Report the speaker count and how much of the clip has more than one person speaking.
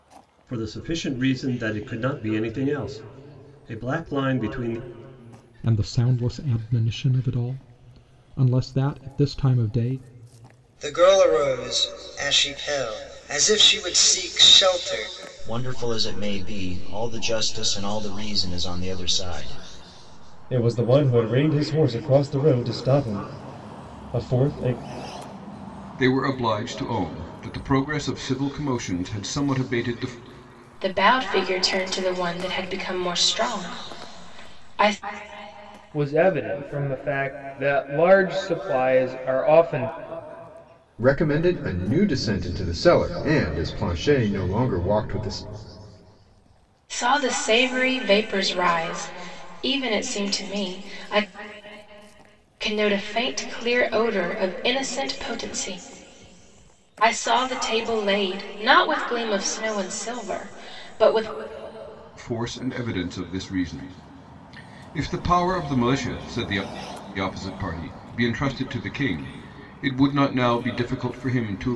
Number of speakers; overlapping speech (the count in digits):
9, no overlap